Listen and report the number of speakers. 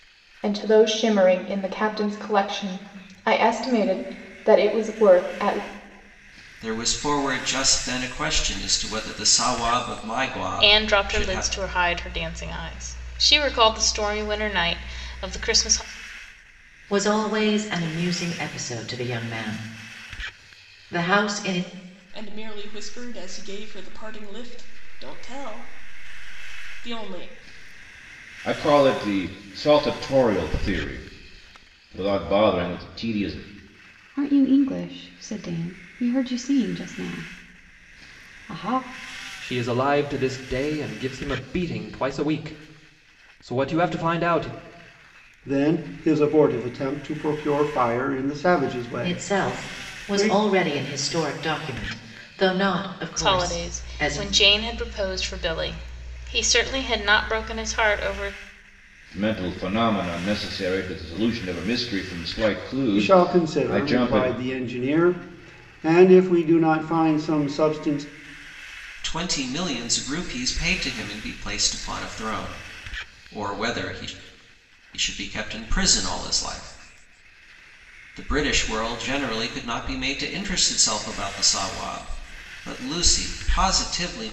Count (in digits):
9